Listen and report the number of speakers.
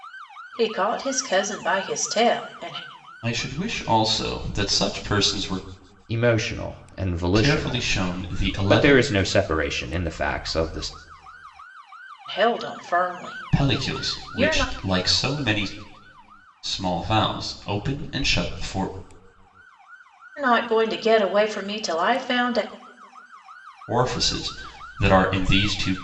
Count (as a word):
three